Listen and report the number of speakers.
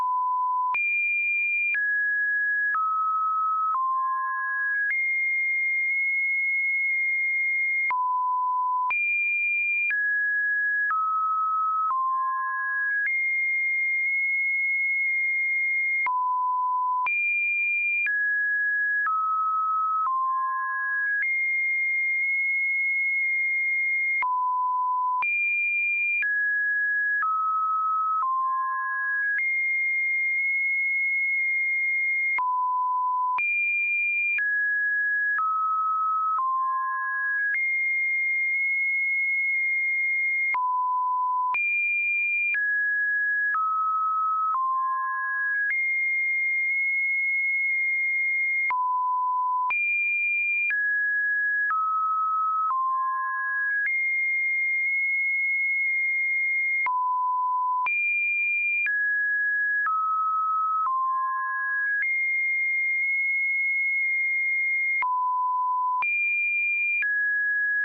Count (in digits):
0